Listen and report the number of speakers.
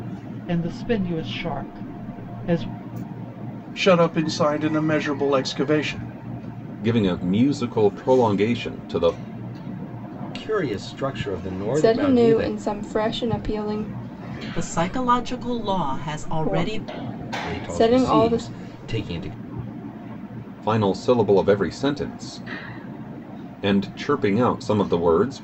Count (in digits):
6